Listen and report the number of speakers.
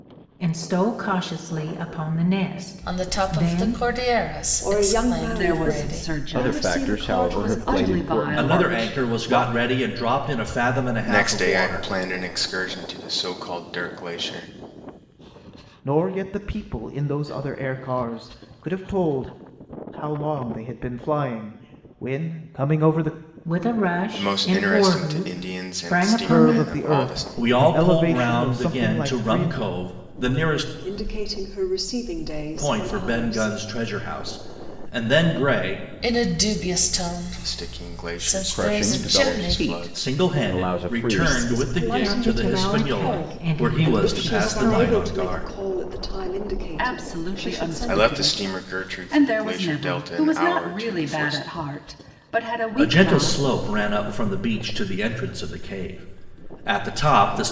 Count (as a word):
eight